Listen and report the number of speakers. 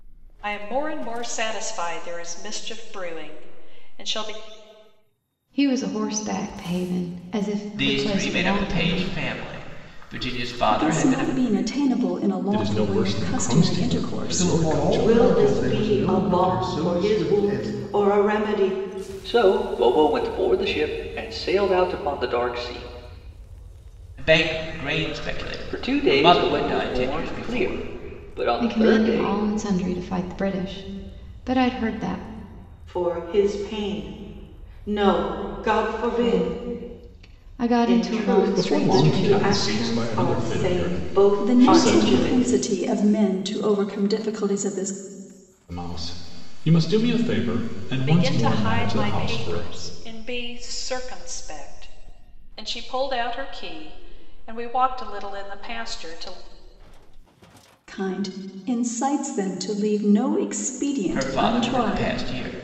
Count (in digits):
8